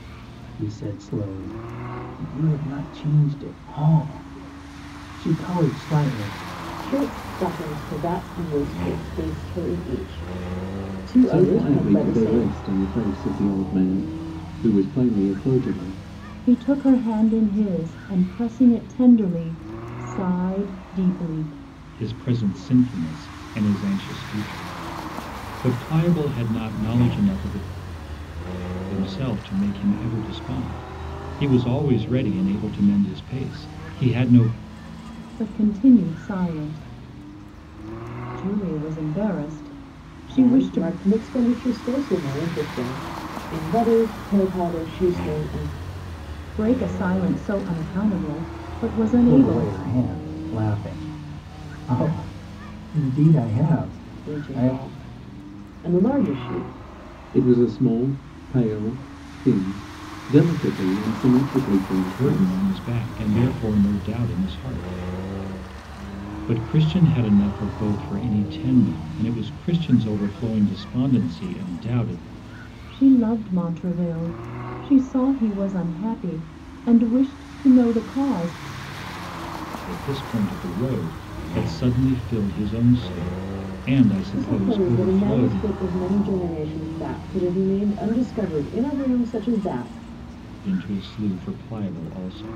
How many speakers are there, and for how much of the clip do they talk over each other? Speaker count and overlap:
five, about 6%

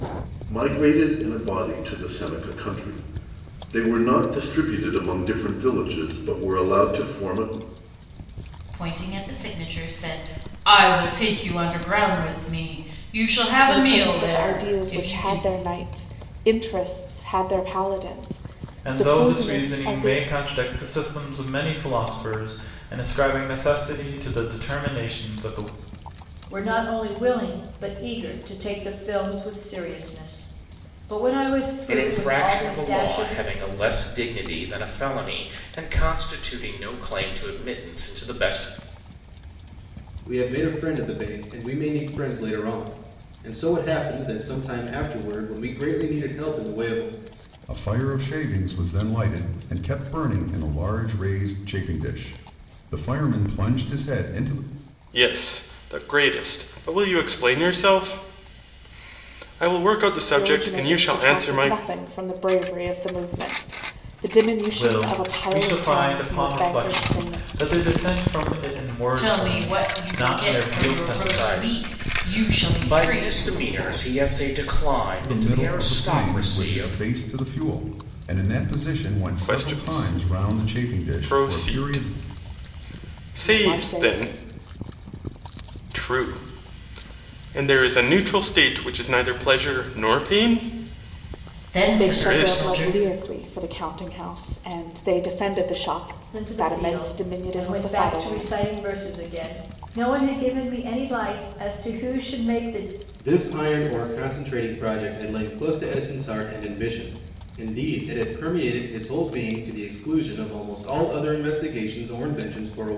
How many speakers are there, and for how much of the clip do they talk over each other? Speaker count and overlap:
nine, about 20%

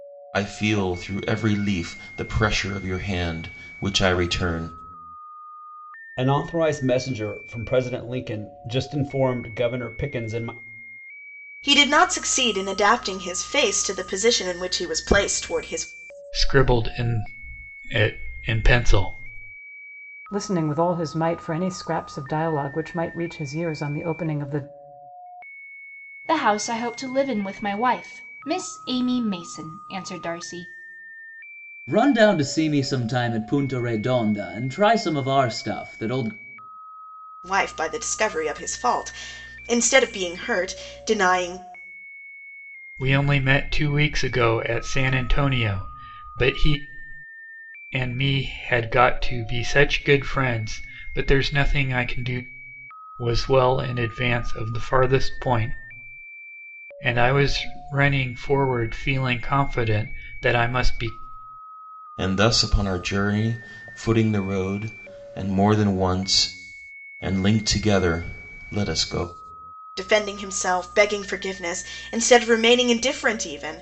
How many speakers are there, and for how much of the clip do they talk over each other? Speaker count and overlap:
seven, no overlap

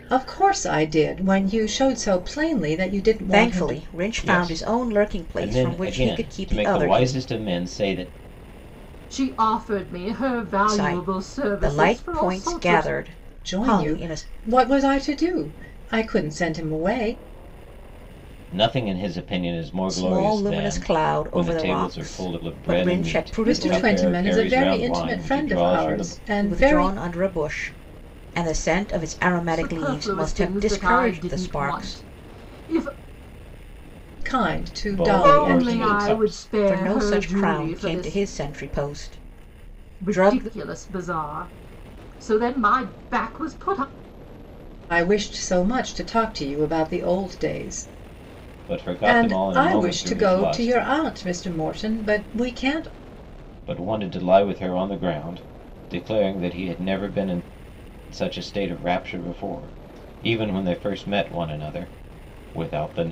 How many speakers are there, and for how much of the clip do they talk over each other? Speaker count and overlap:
four, about 34%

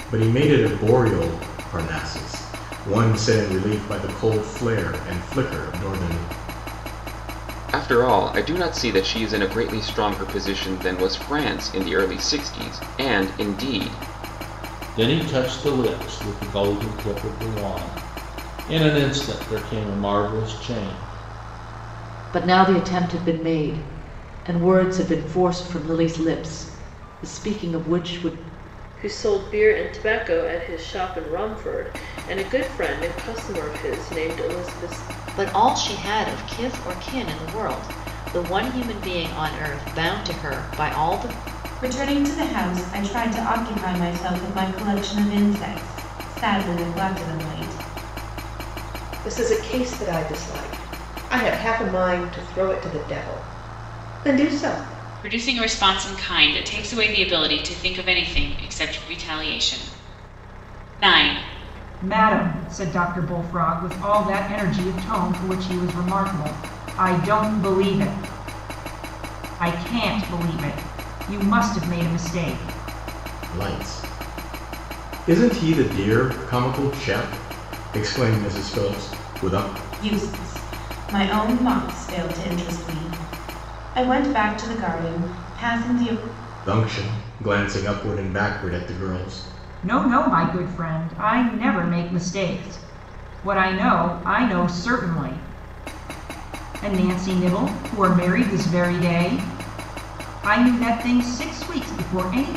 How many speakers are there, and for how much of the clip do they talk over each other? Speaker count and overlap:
ten, no overlap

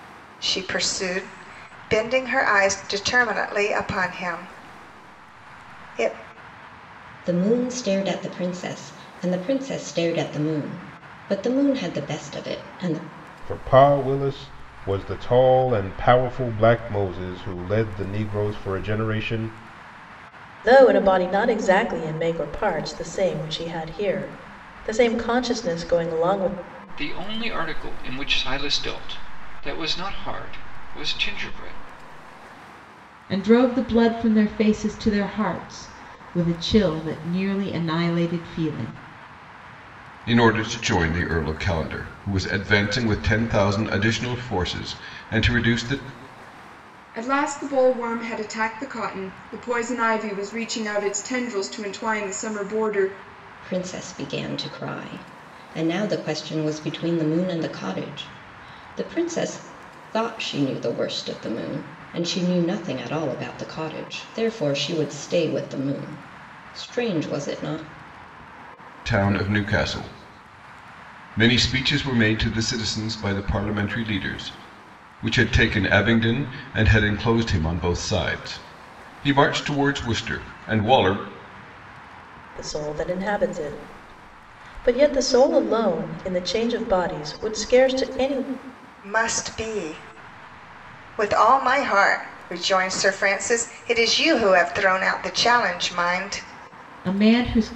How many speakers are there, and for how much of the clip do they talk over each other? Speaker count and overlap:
eight, no overlap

